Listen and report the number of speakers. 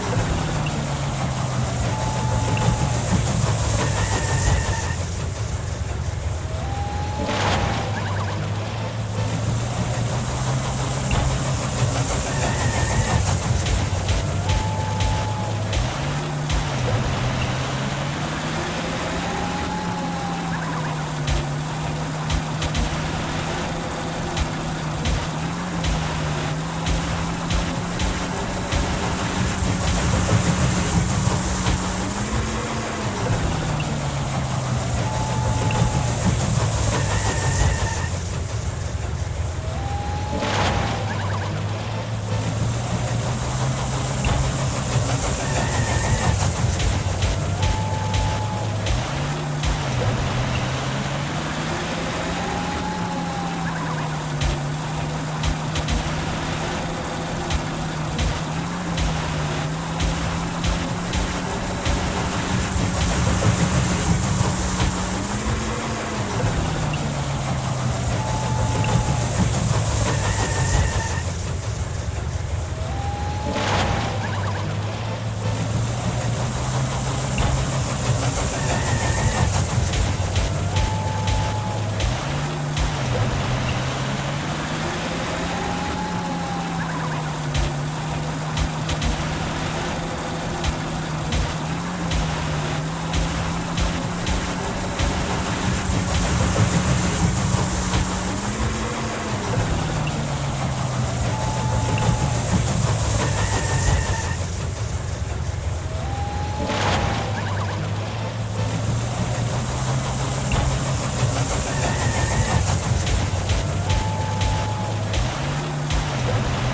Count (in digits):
0